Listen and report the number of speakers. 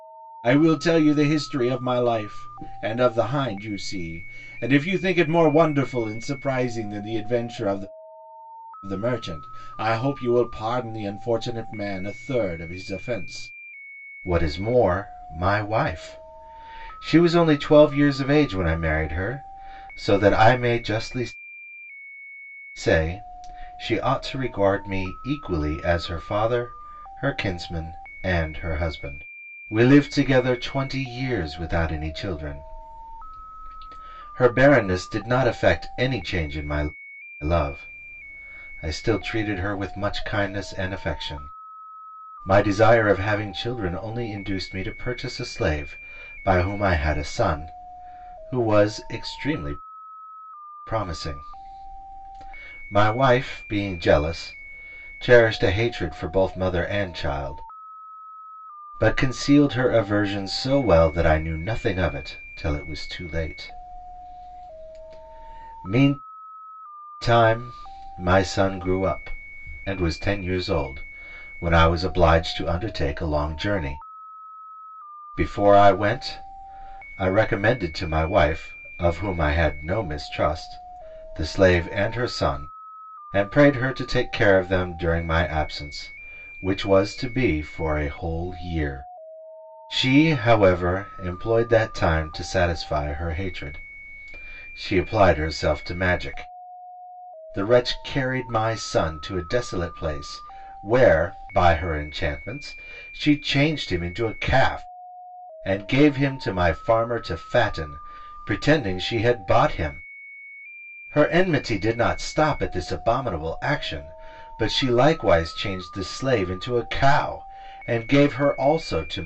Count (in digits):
1